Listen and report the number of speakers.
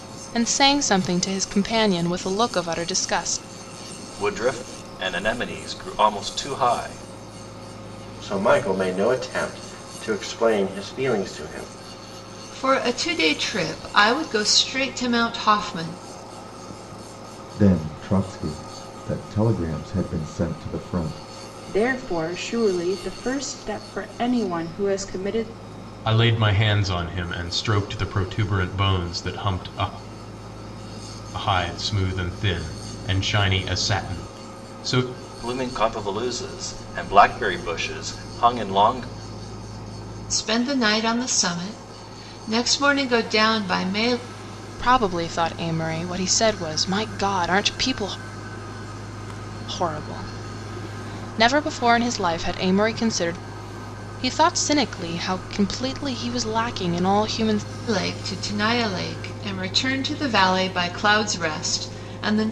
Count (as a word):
seven